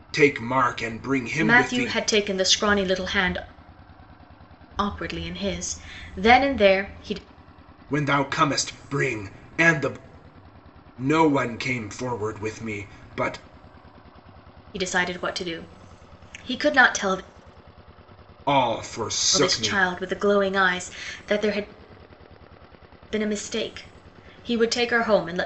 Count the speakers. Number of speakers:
2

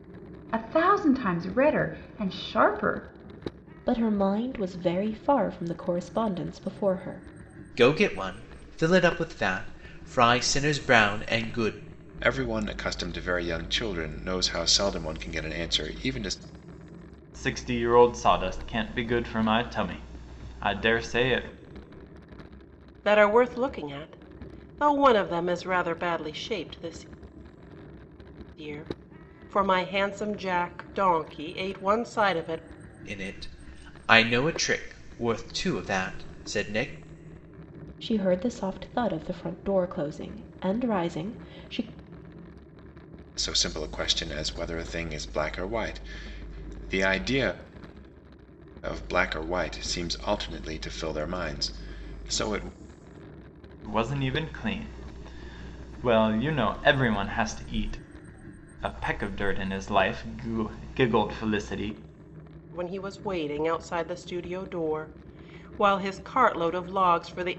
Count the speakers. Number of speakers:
6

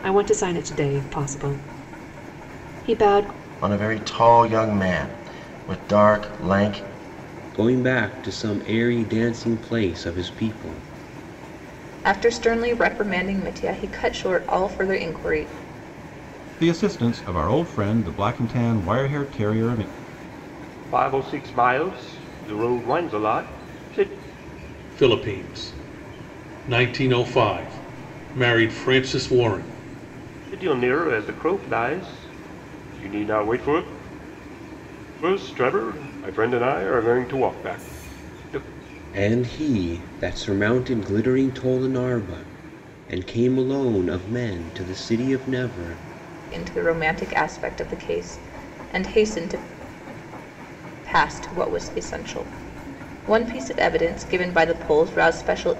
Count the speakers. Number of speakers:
7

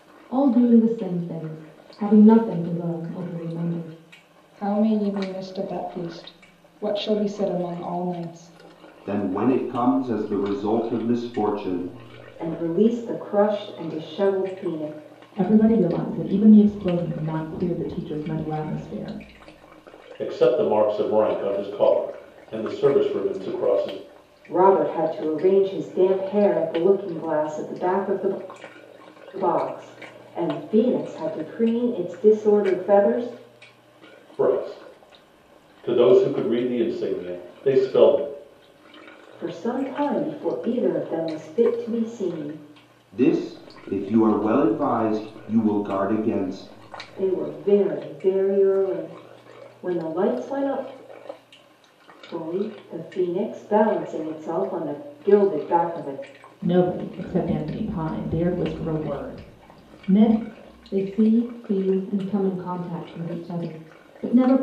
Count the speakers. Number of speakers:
6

